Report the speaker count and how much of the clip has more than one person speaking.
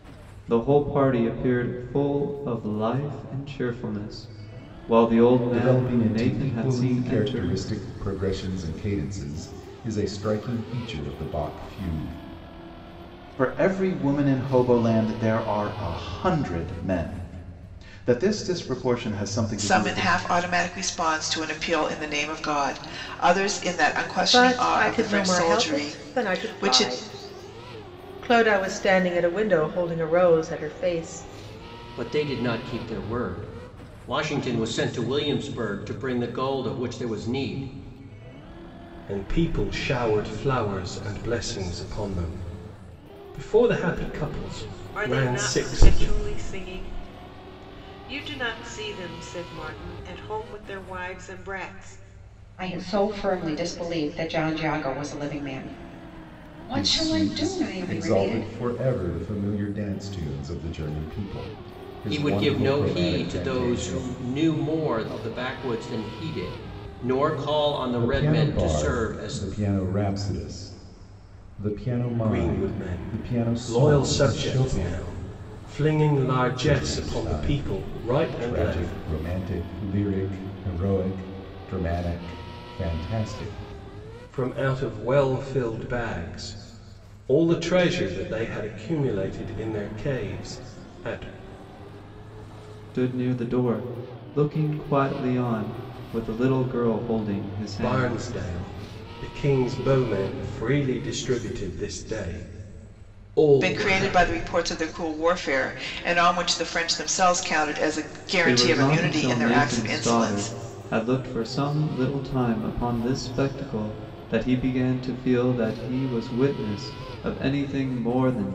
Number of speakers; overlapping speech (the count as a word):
nine, about 18%